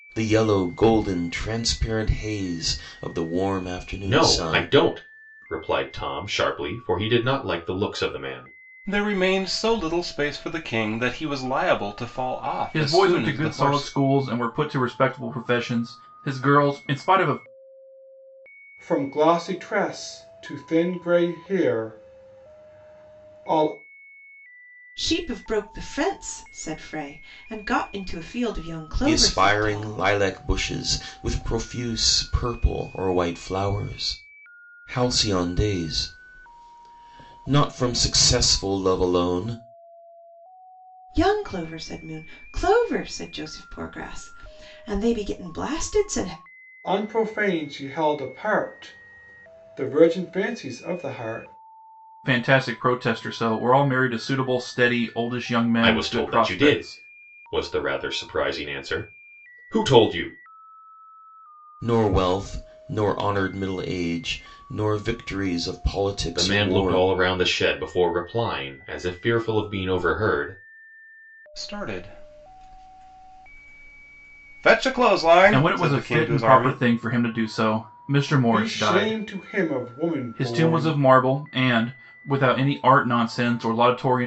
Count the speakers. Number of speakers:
6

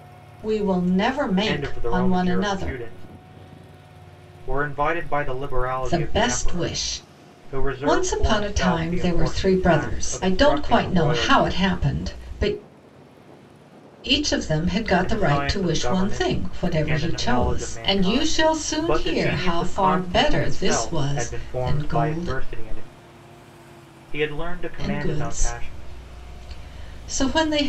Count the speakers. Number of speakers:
2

